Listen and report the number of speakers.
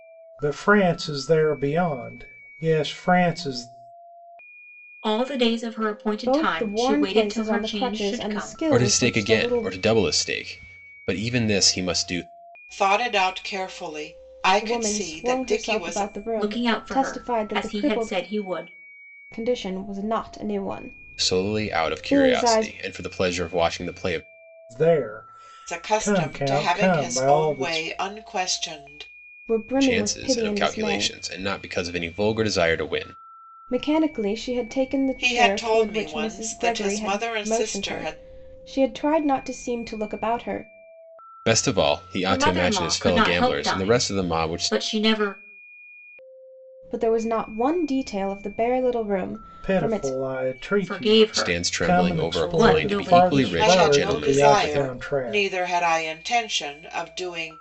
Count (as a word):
five